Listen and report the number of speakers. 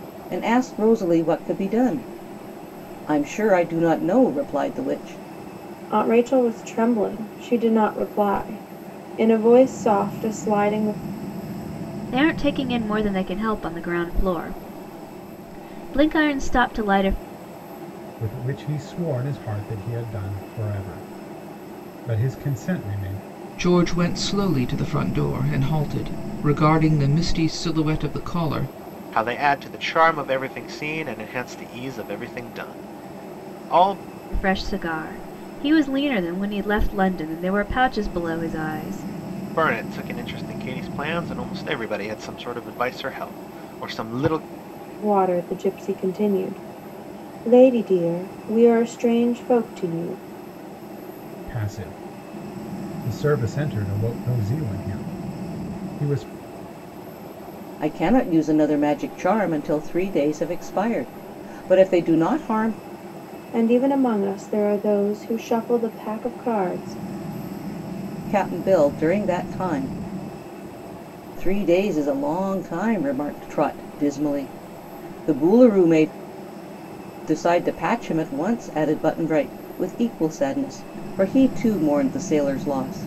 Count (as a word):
six